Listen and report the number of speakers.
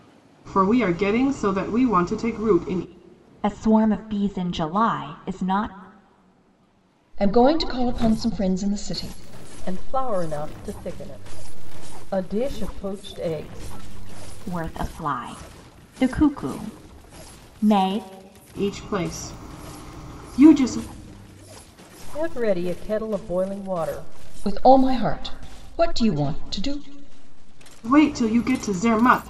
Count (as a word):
four